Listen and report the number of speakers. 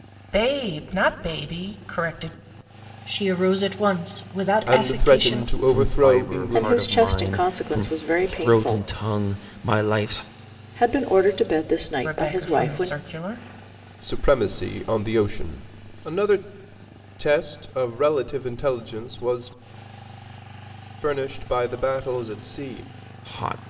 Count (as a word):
five